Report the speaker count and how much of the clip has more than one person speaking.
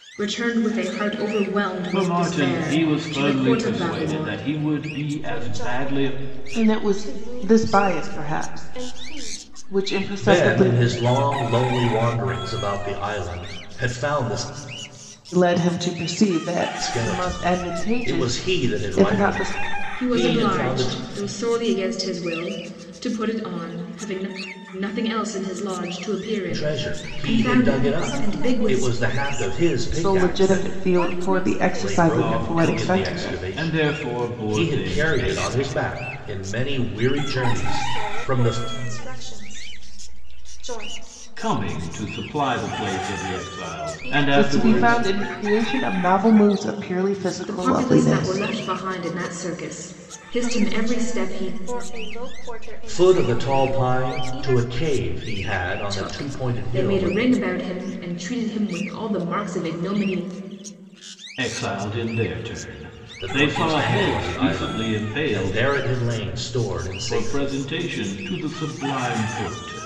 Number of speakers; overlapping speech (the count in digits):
5, about 44%